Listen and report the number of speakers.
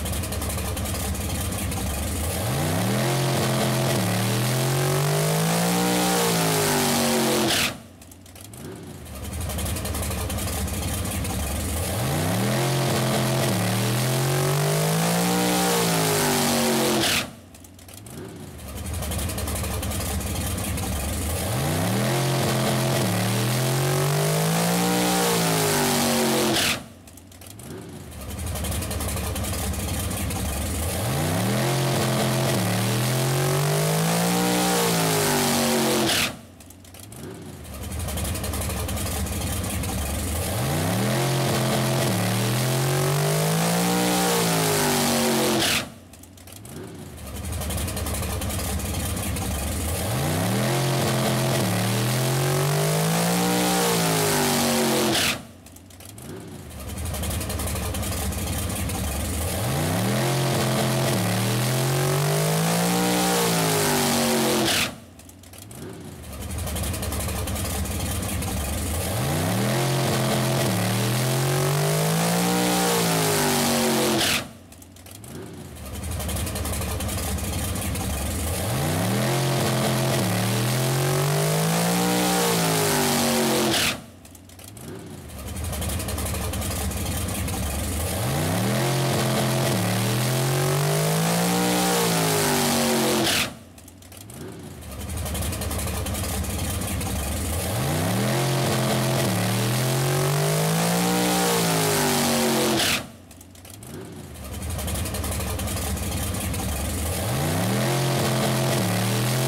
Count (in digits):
0